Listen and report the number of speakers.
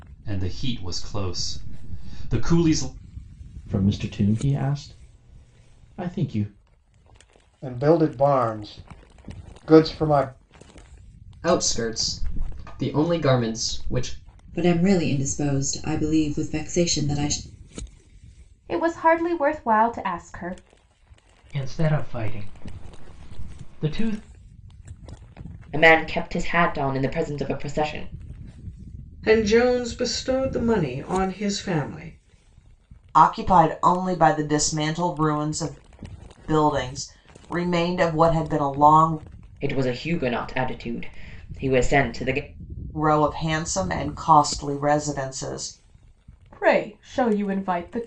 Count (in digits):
10